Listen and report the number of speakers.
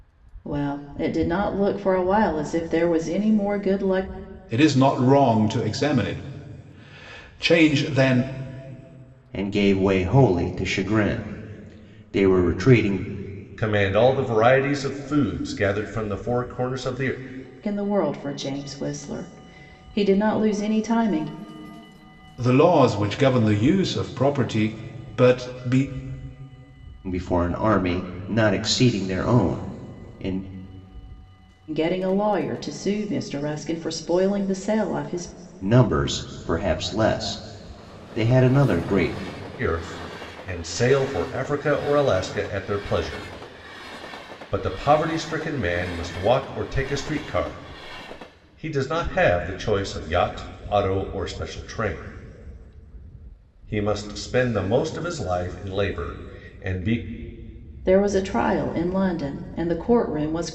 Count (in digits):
4